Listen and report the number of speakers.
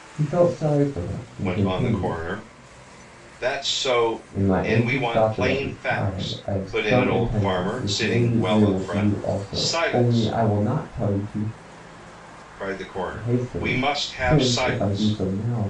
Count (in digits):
2